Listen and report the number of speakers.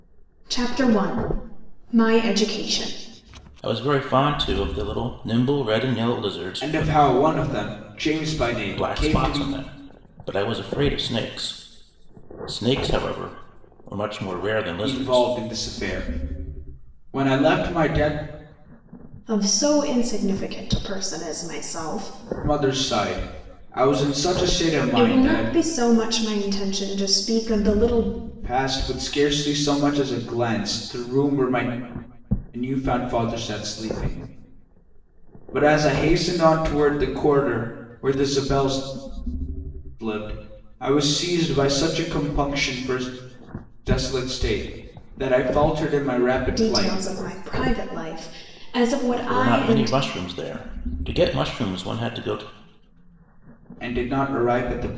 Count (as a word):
three